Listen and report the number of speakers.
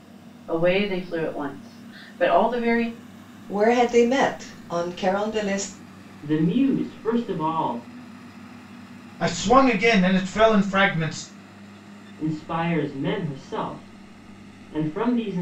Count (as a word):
four